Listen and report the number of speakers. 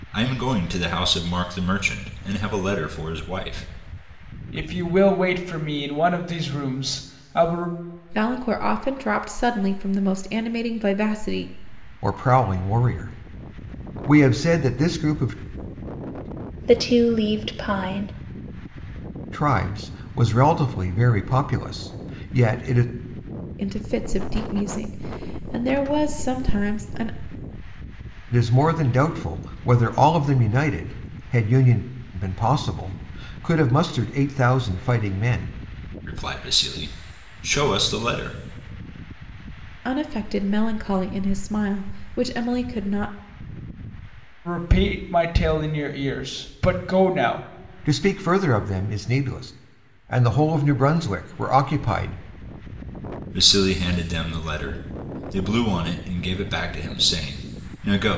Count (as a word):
five